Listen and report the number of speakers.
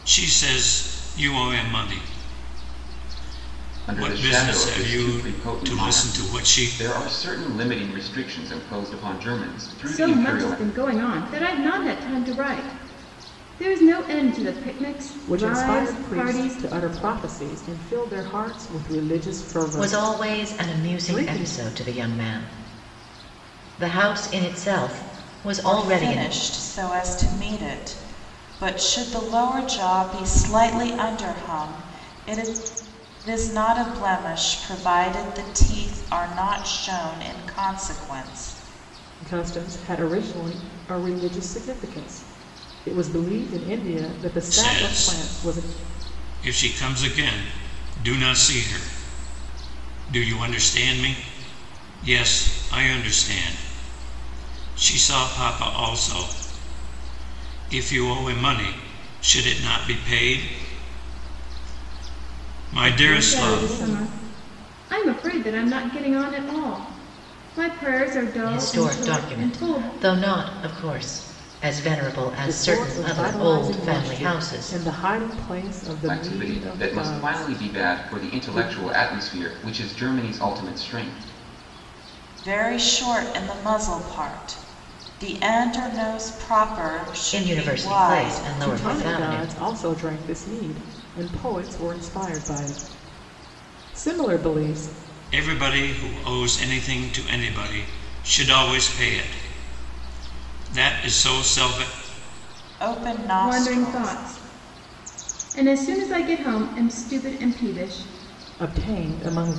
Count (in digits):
6